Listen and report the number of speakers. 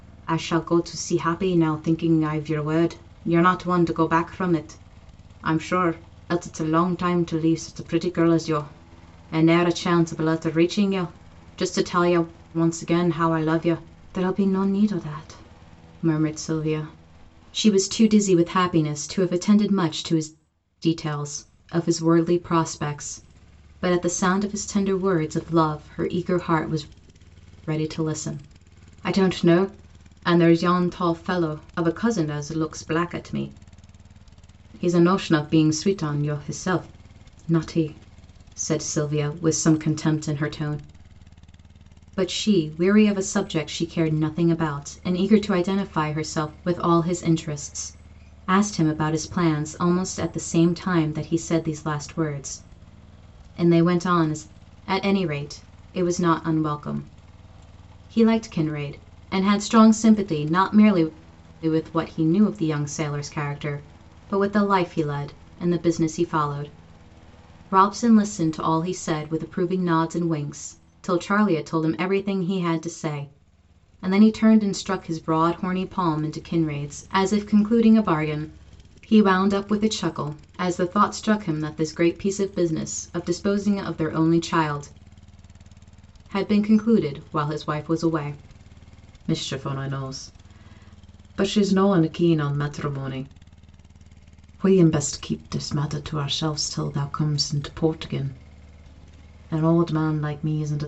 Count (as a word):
one